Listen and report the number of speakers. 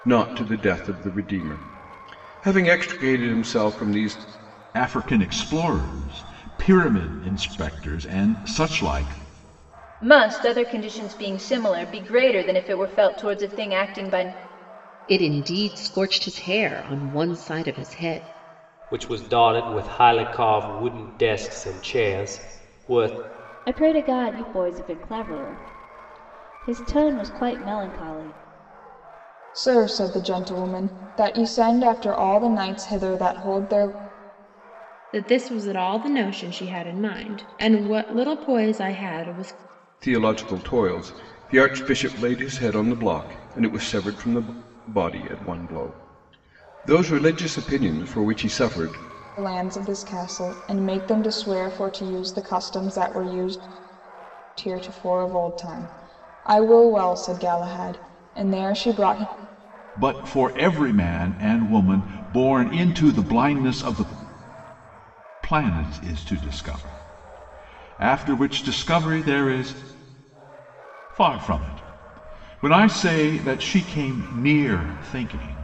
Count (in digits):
8